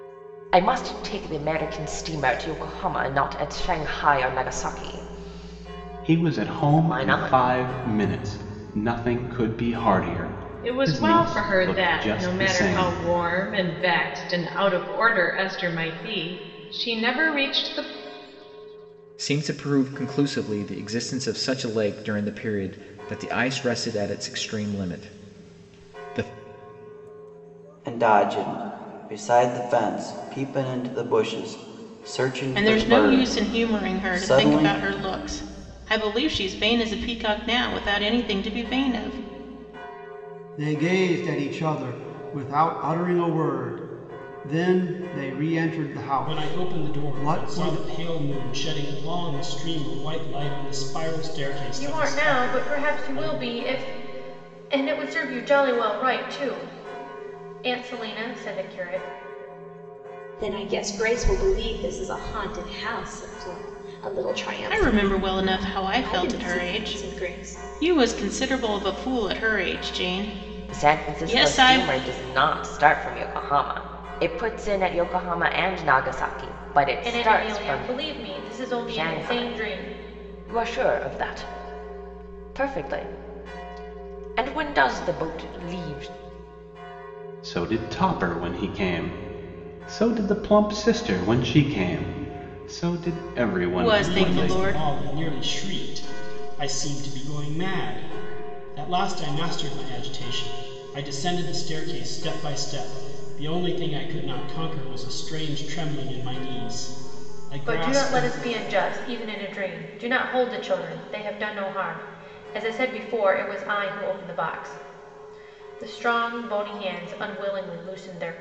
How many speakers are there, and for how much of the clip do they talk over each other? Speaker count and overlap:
10, about 15%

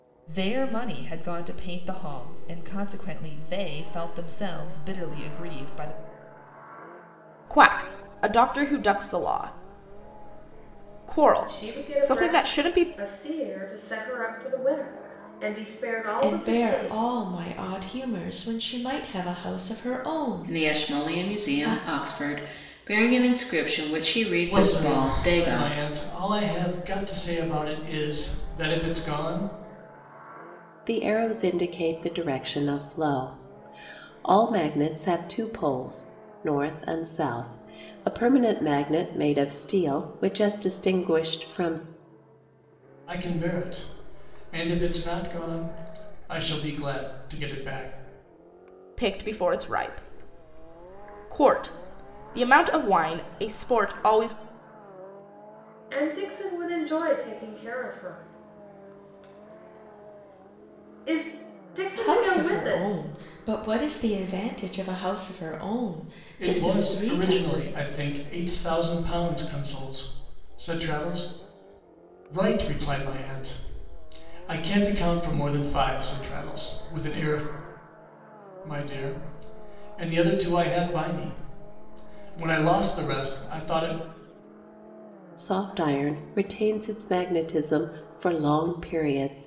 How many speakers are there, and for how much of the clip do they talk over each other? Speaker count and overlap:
7, about 8%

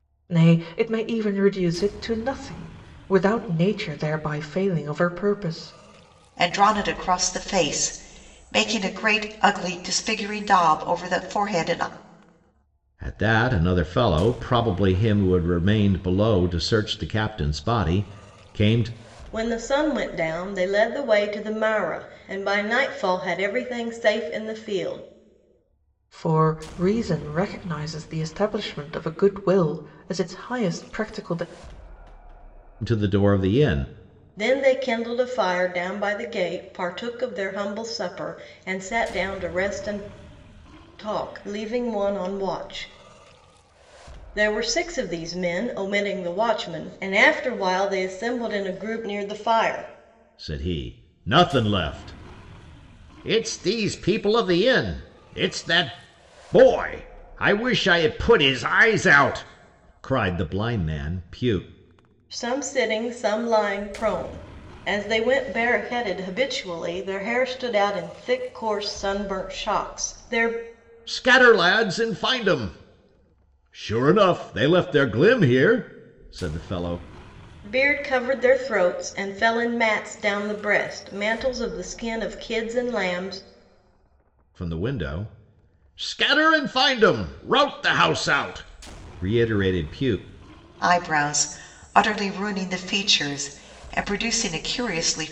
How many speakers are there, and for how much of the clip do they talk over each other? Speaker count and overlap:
4, no overlap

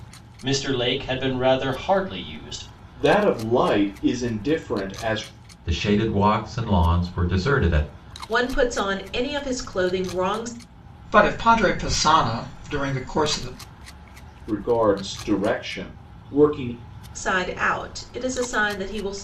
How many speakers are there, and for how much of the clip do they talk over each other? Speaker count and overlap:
5, no overlap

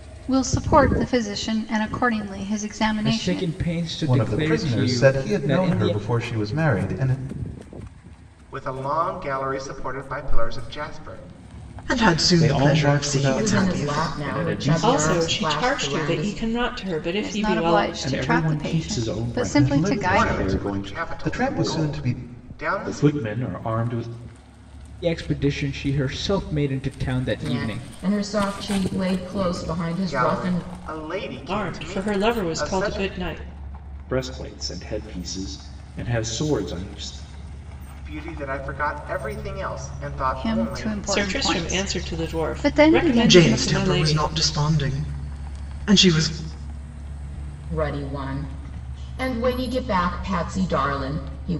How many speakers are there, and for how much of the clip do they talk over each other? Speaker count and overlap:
8, about 36%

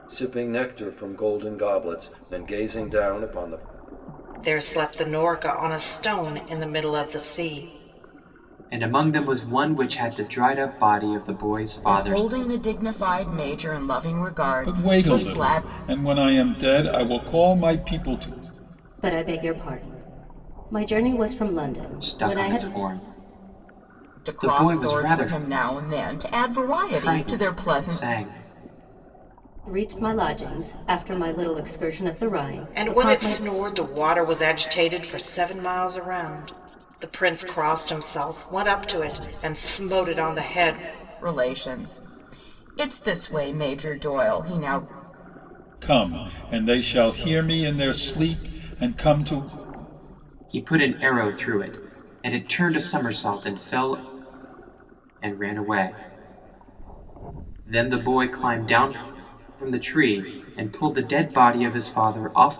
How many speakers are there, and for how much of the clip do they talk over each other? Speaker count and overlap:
6, about 9%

